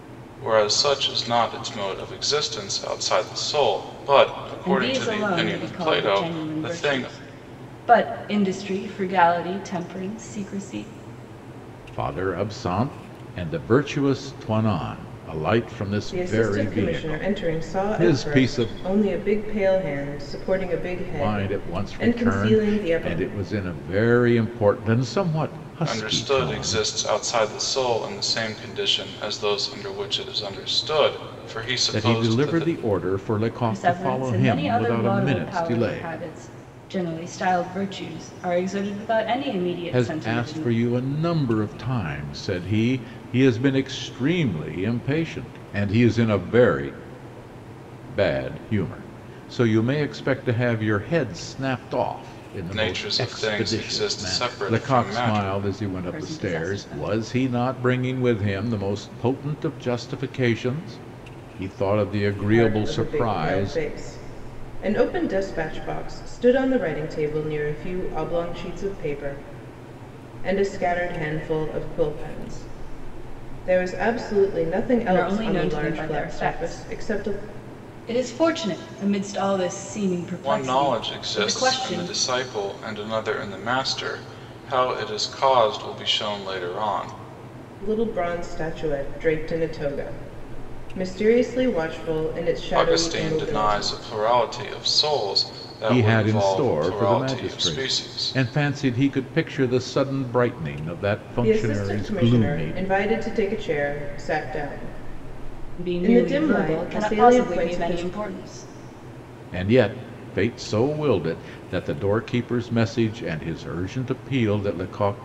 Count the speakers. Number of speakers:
4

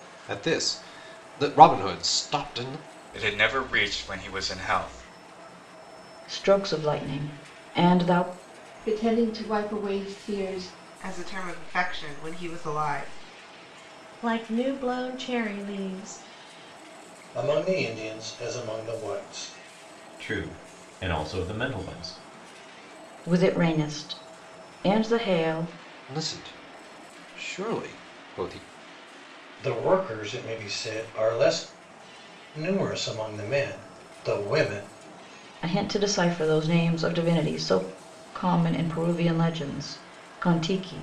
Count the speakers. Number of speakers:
8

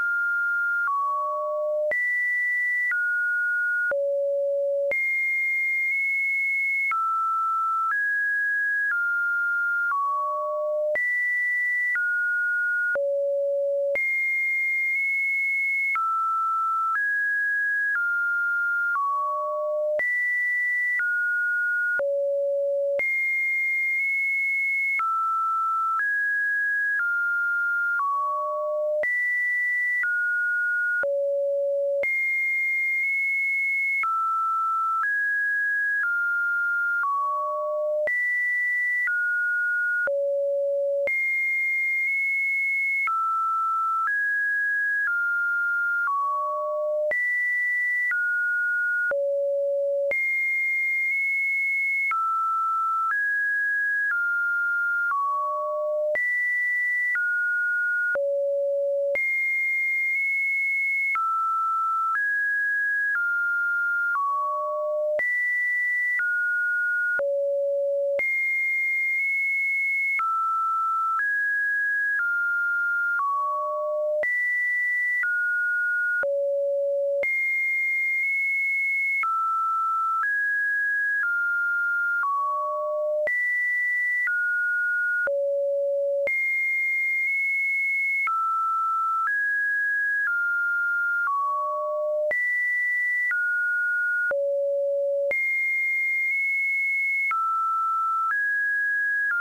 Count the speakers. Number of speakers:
0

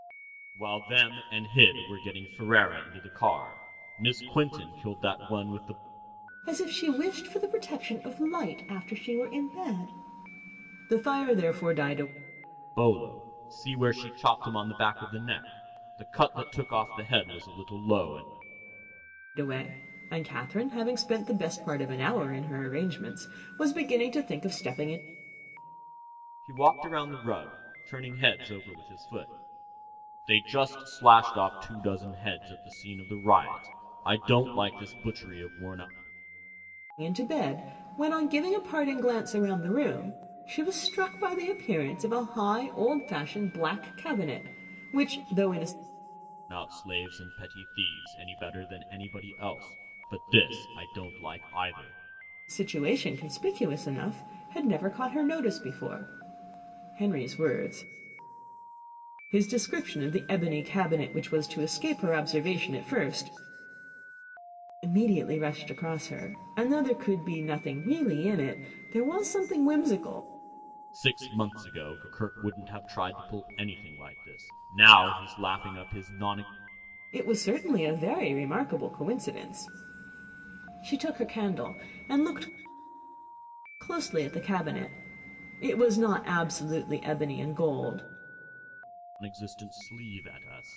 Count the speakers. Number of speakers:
2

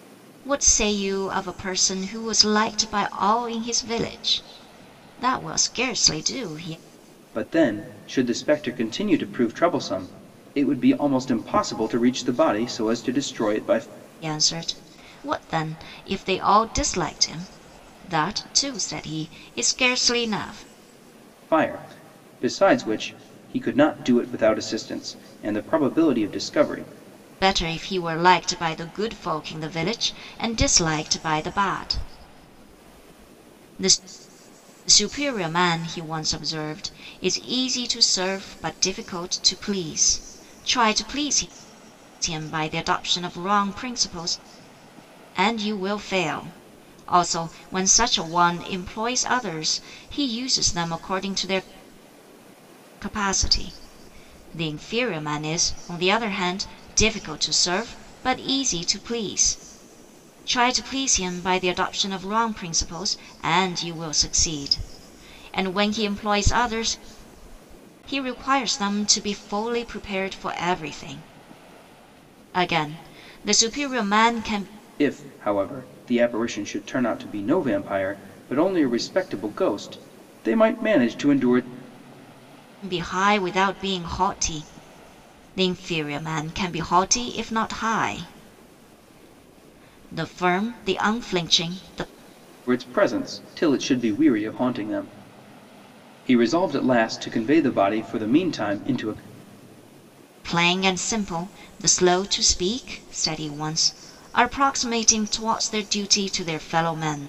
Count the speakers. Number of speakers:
2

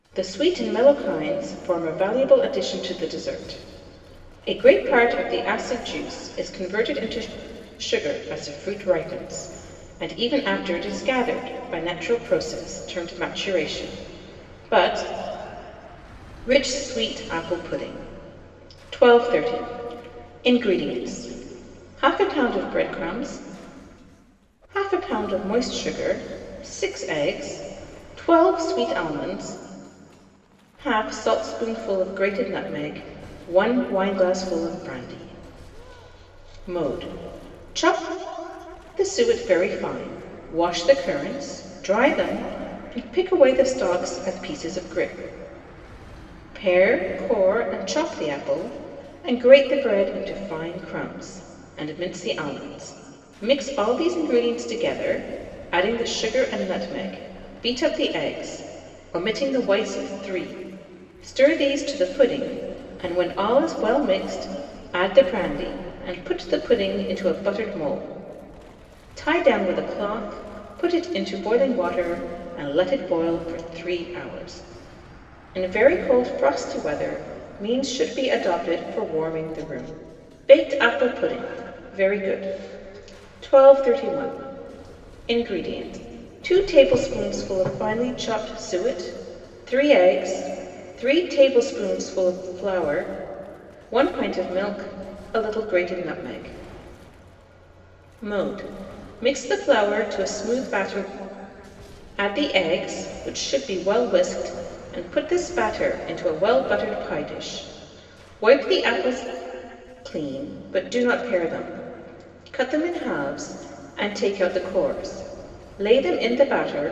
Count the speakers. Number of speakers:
1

